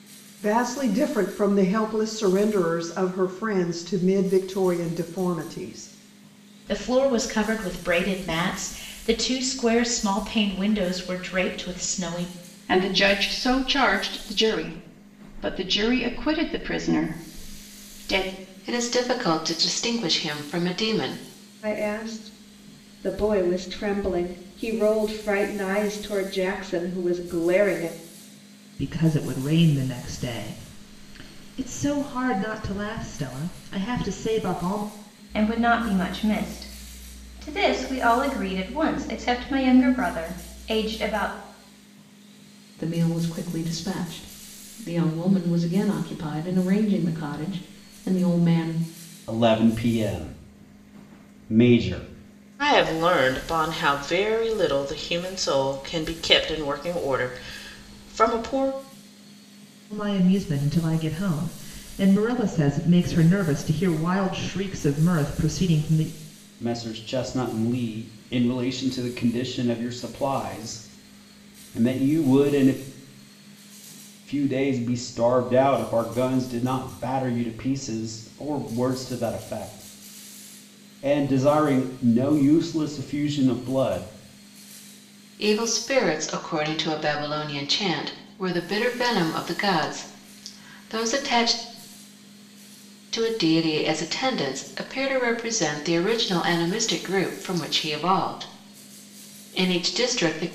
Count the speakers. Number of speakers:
10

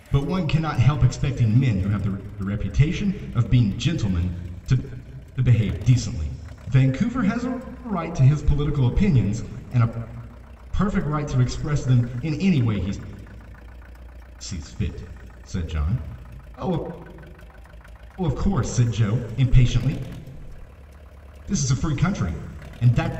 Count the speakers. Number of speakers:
1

